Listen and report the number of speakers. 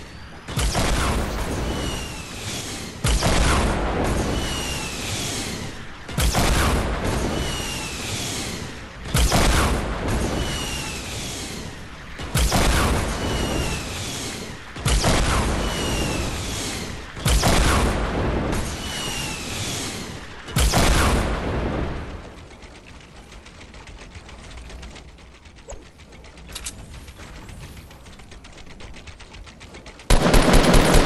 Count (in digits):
0